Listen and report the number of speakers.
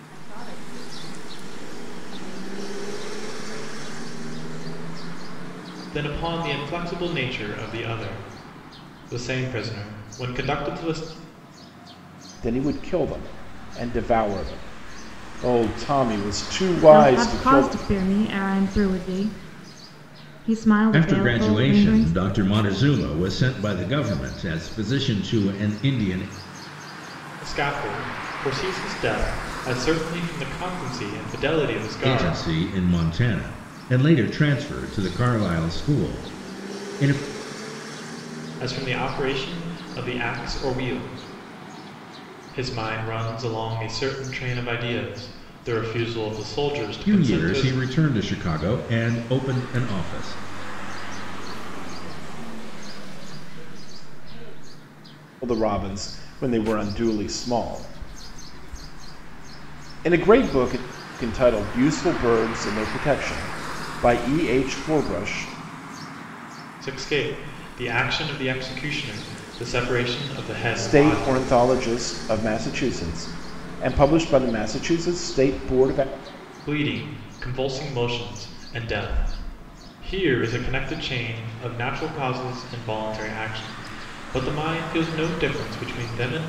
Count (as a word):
five